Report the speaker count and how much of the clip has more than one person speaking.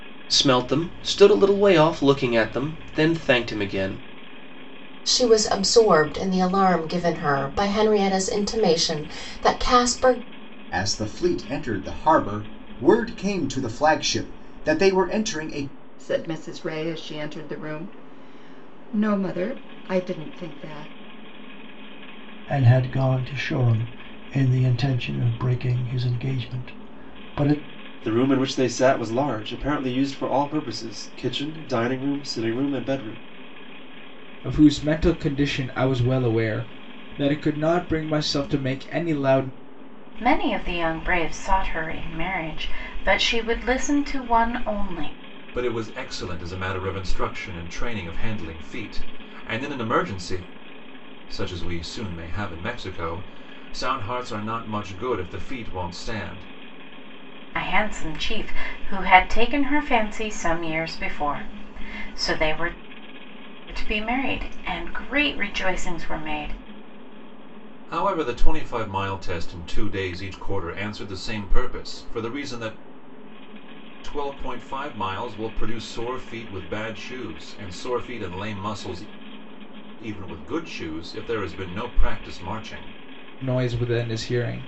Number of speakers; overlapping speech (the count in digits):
9, no overlap